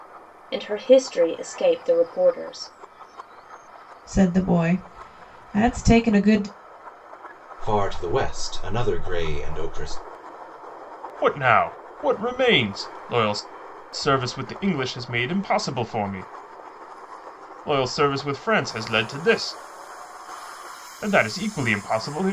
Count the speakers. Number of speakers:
4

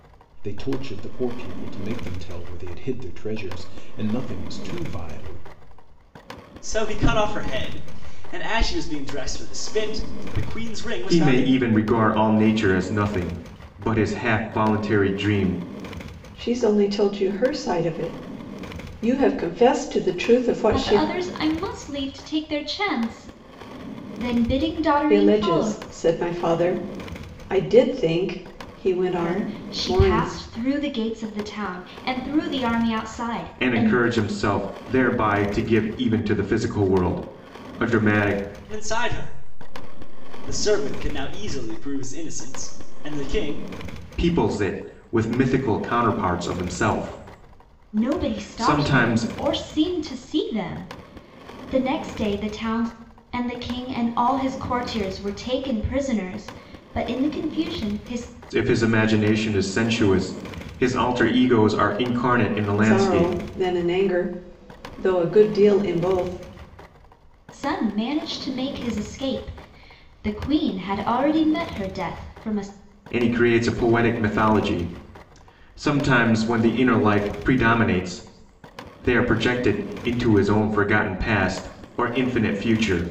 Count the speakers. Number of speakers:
5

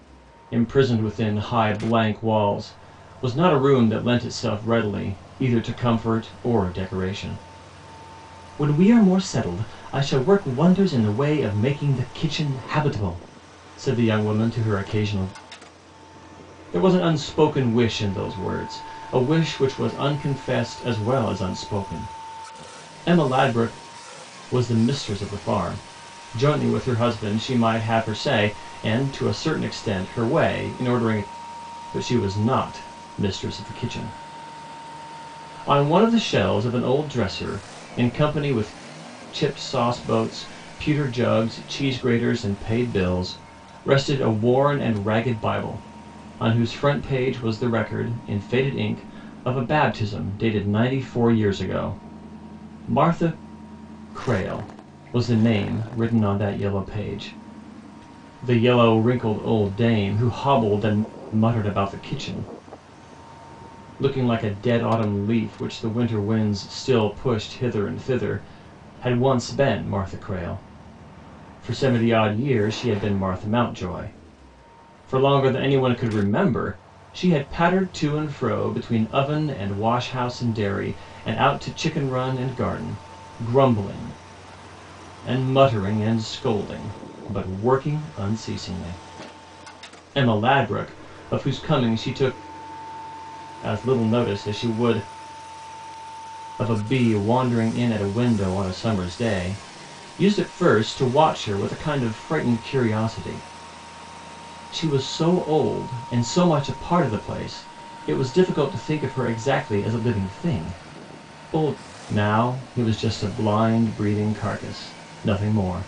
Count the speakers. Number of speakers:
1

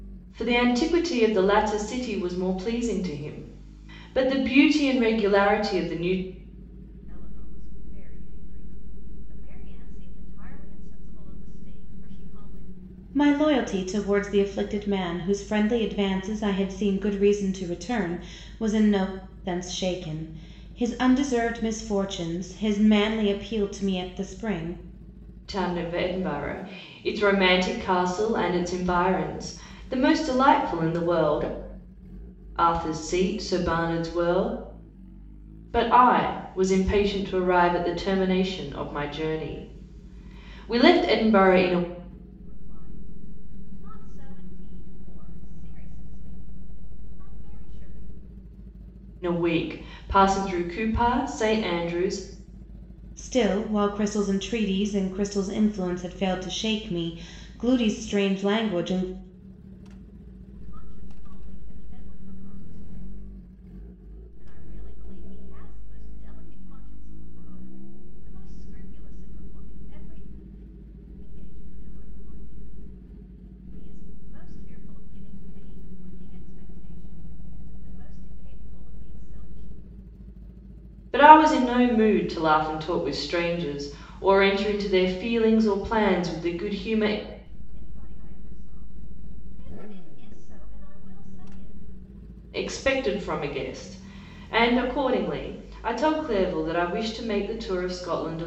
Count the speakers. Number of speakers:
3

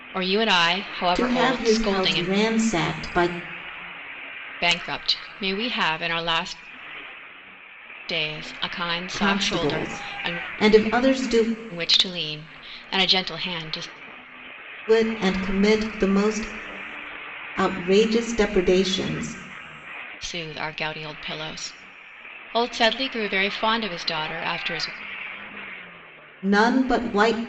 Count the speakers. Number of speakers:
2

